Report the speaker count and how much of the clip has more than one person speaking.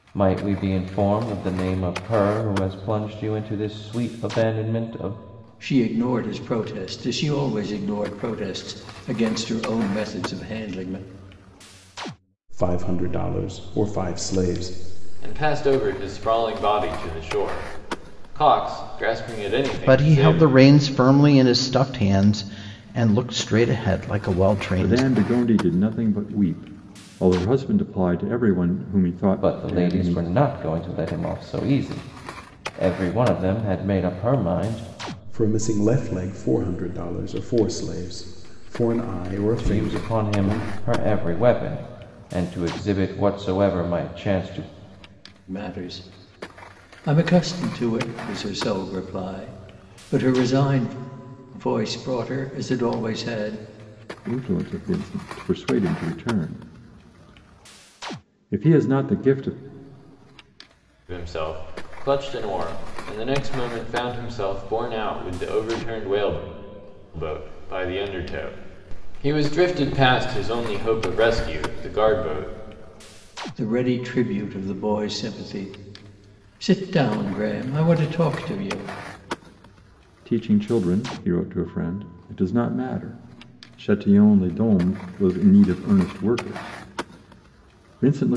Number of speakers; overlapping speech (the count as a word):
six, about 4%